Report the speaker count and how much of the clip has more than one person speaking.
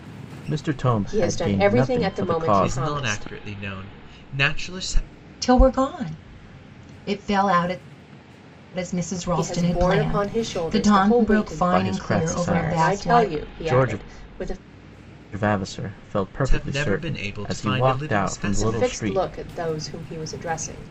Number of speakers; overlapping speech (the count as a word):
four, about 47%